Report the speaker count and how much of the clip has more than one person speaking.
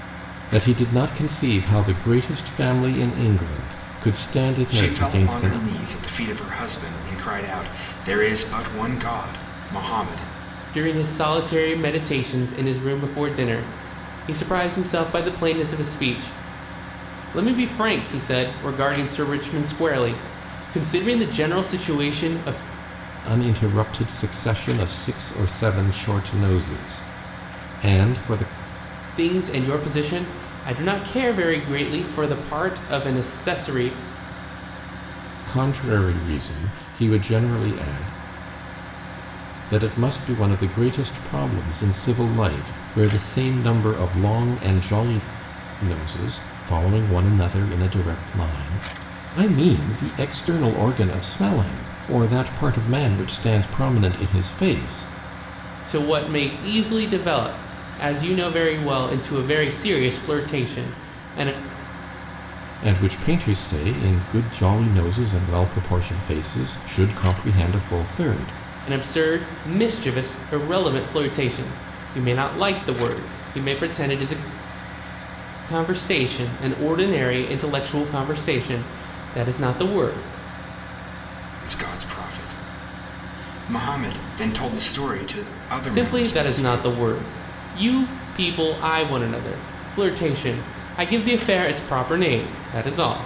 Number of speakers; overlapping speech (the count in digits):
3, about 2%